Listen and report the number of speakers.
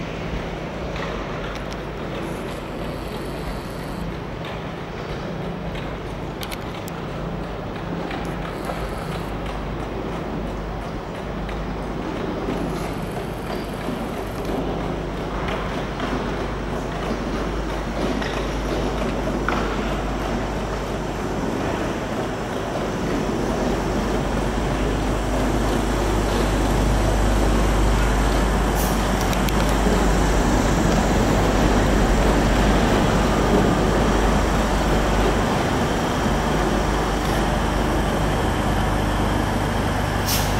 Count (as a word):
zero